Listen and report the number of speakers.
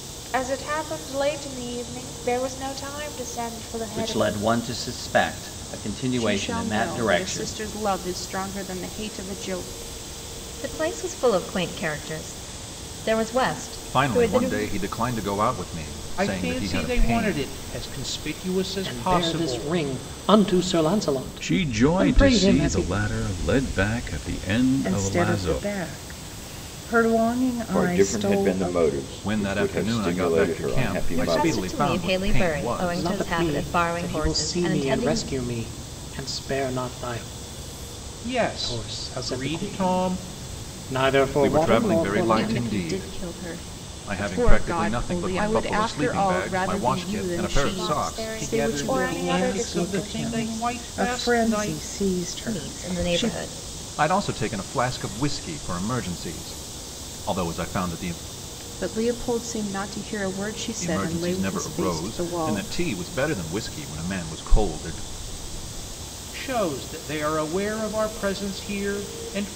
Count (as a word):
ten